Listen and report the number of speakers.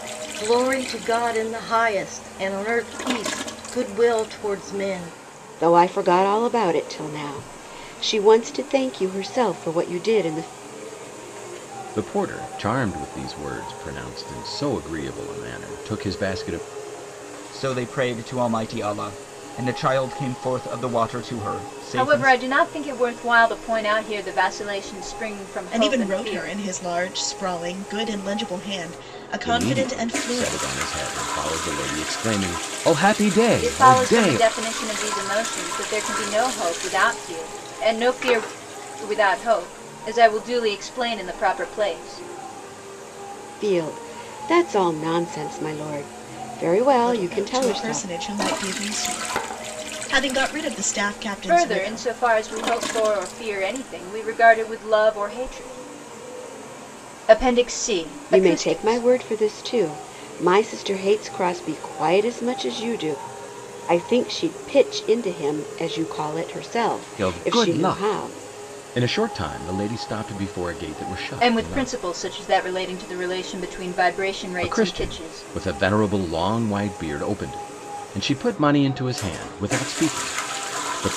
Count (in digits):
6